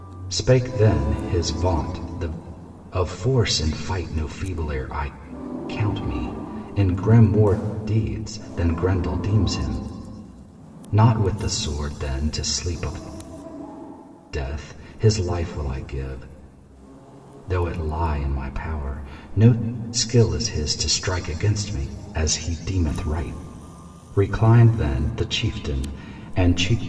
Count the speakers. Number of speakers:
one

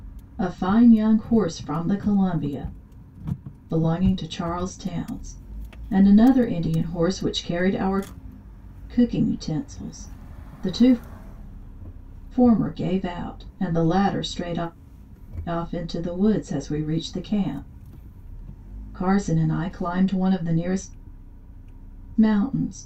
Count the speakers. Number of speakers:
one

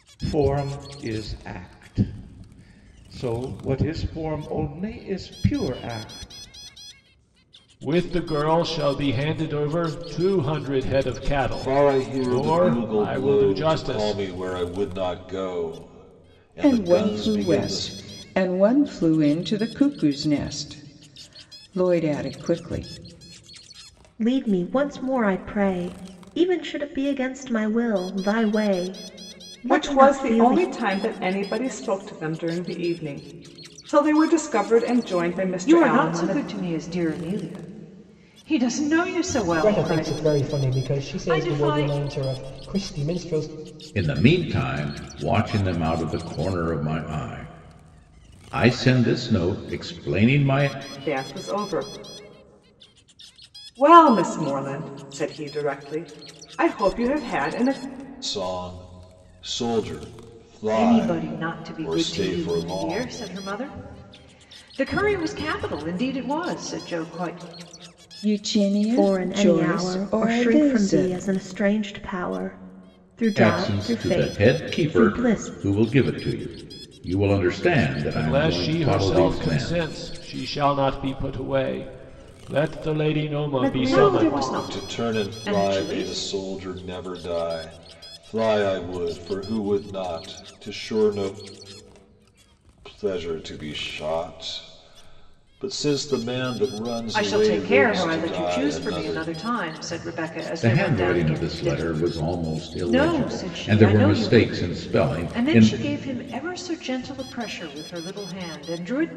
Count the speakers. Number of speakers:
nine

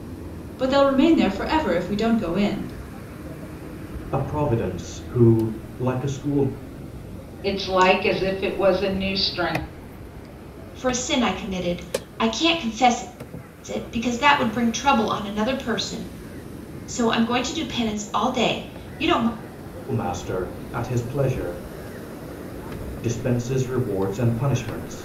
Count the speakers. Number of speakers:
four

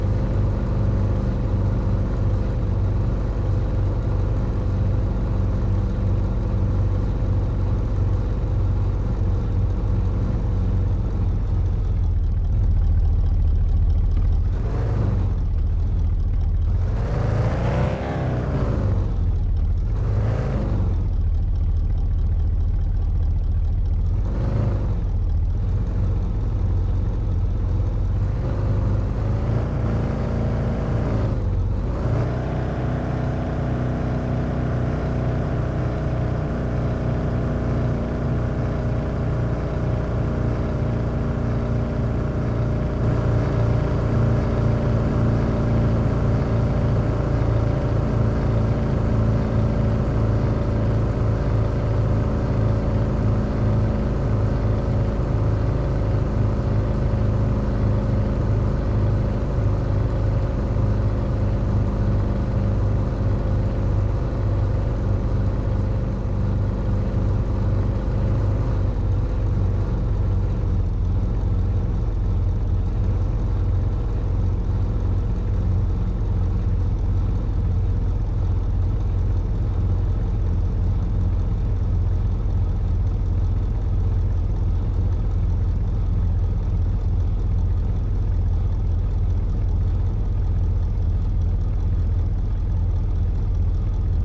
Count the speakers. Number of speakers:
zero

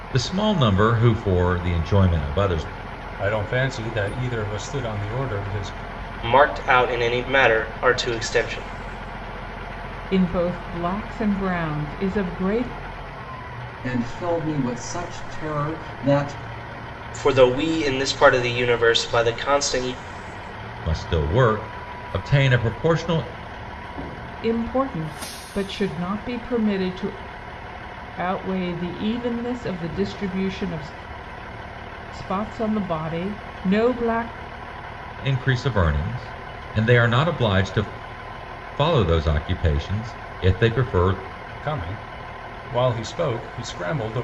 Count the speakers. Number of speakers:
five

